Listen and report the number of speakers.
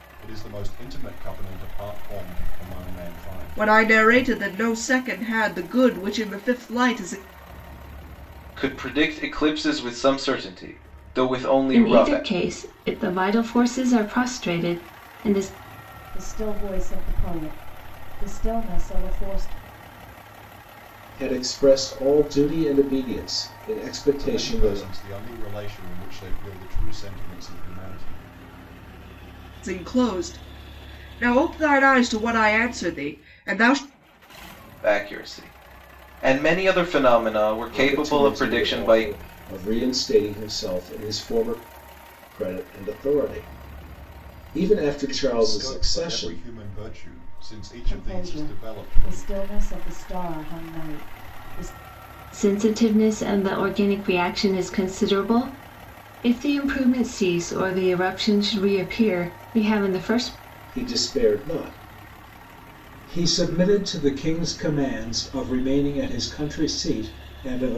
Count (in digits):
6